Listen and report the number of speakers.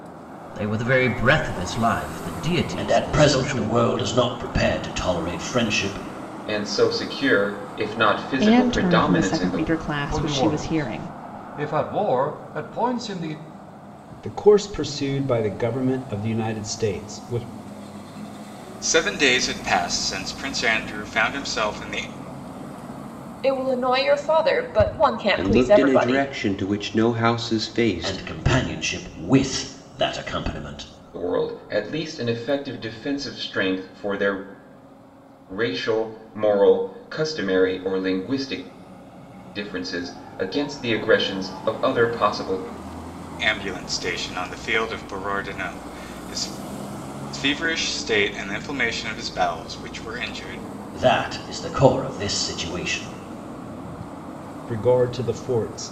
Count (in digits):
9